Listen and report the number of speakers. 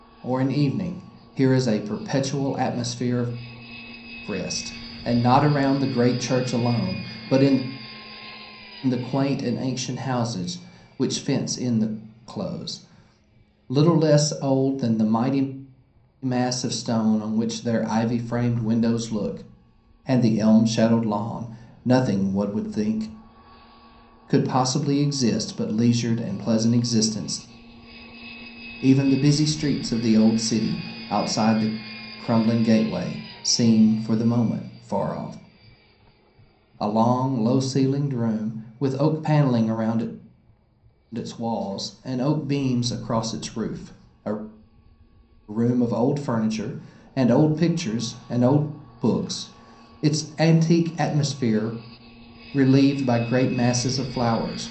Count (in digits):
1